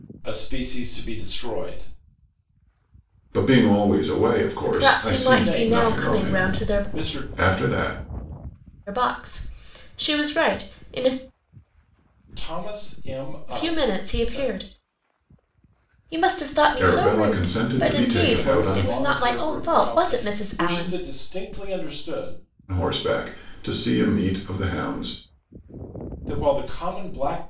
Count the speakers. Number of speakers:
three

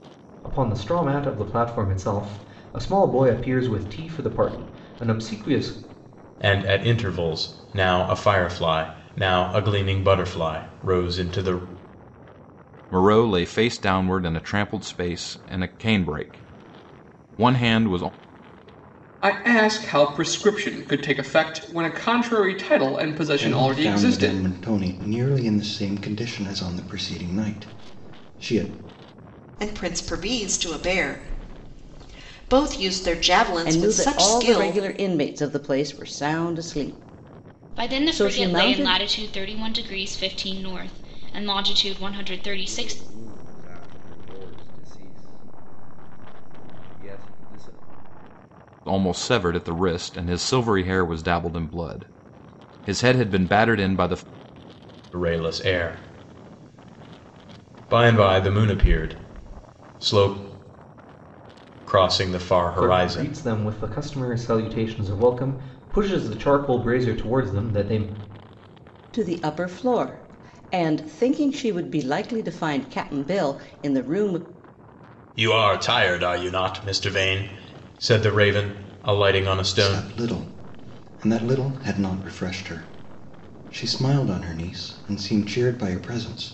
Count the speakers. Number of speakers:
nine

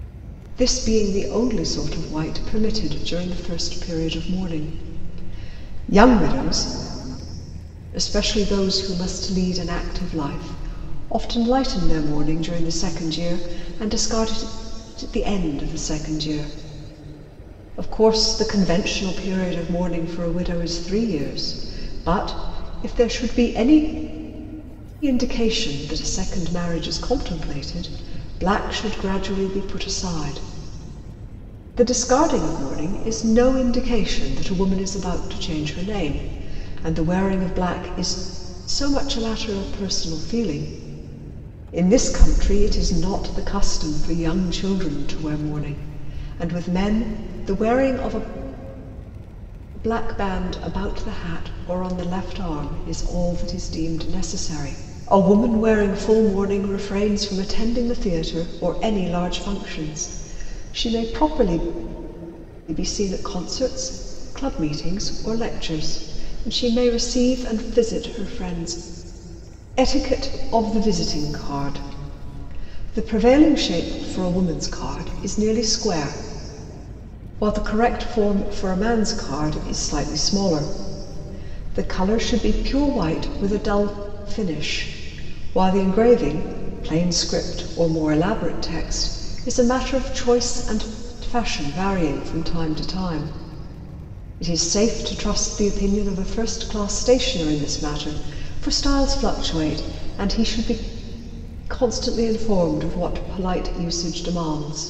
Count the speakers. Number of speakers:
one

